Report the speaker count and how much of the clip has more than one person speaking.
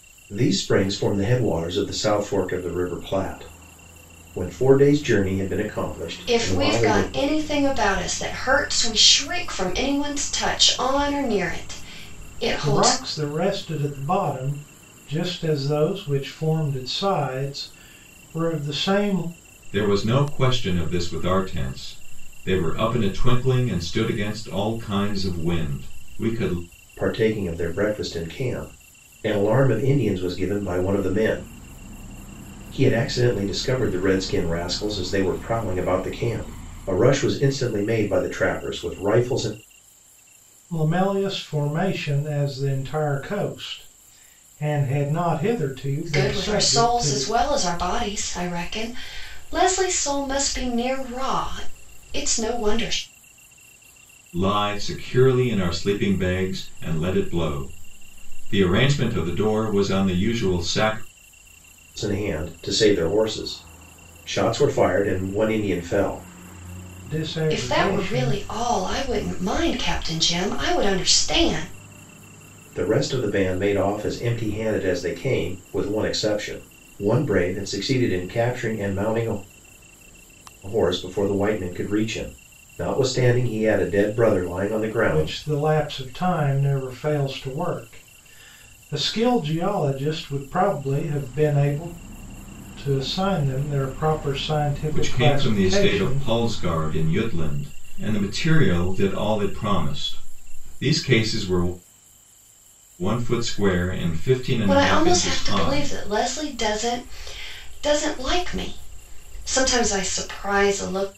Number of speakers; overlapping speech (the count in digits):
4, about 6%